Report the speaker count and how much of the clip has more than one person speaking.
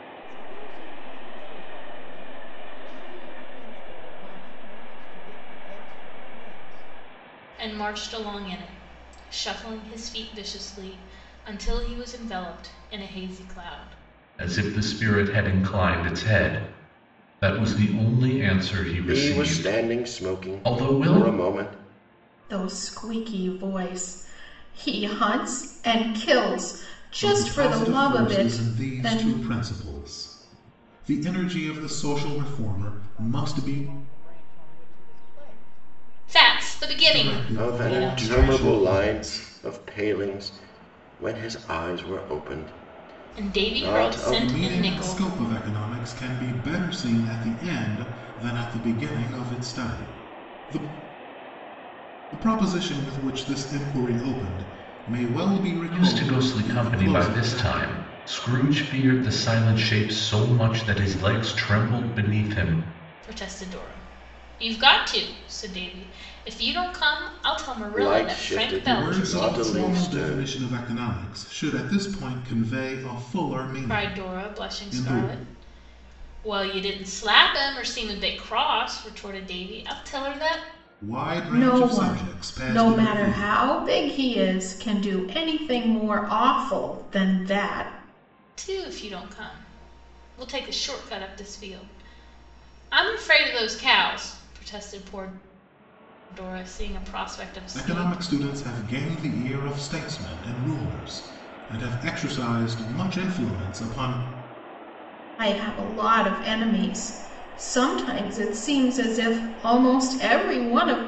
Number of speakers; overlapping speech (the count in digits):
6, about 18%